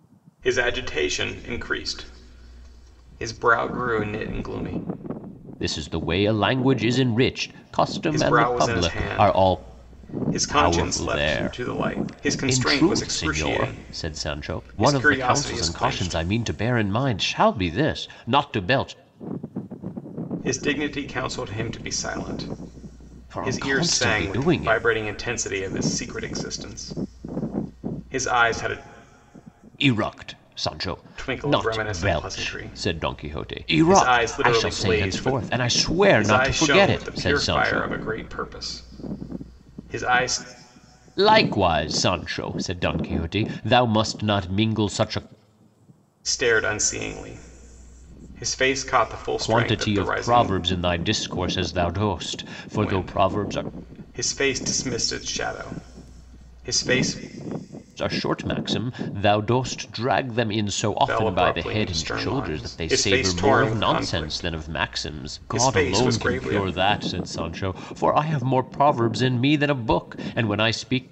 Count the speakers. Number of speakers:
2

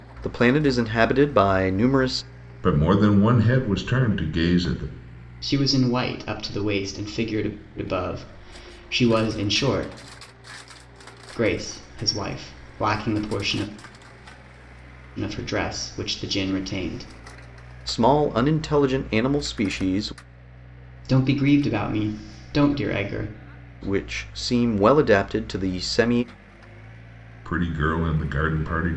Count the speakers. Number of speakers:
3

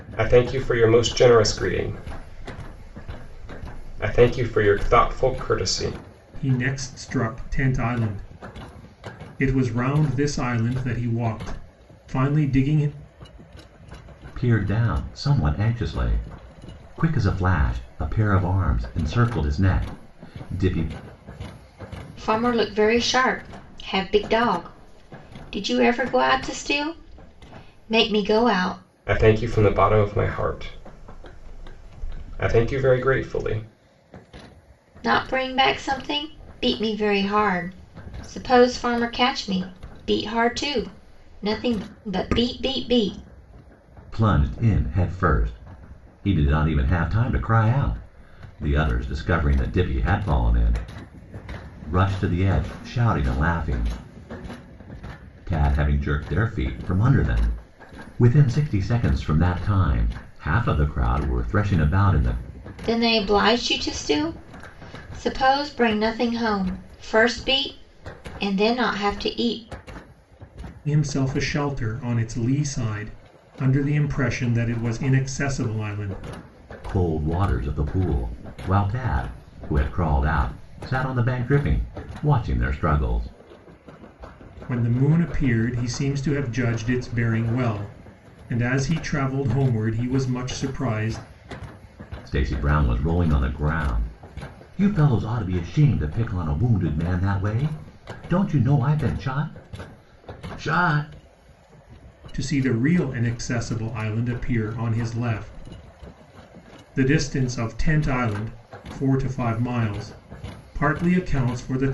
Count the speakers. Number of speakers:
4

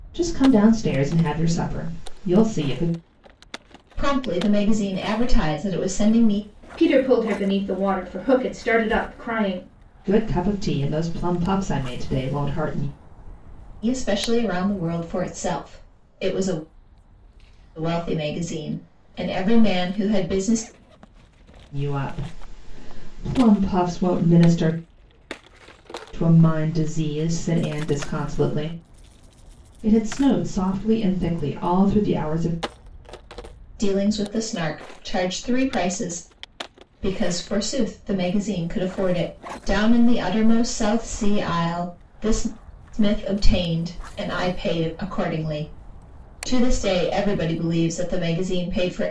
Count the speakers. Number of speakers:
3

